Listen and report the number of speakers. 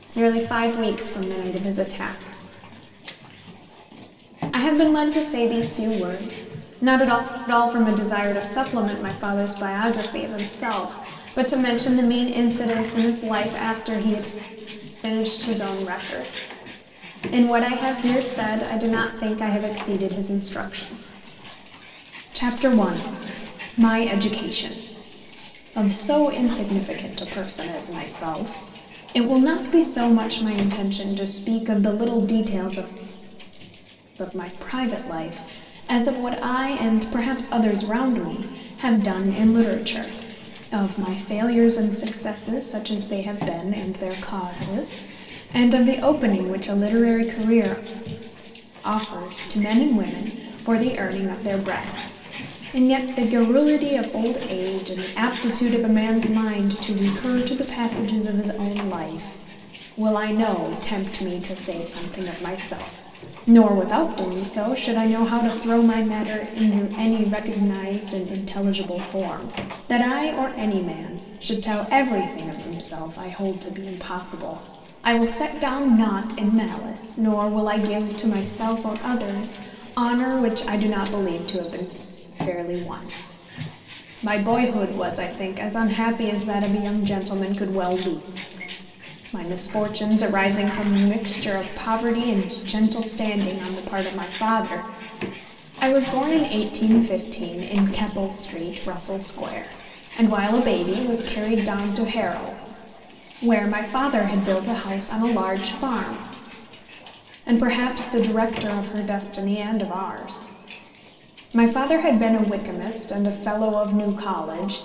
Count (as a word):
one